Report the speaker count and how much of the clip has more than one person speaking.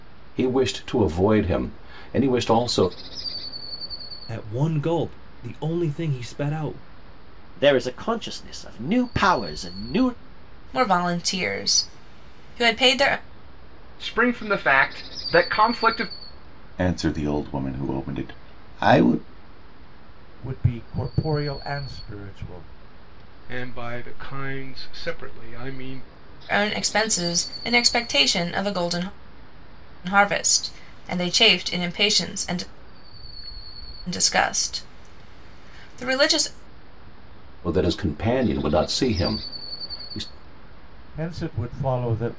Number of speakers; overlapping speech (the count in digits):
8, no overlap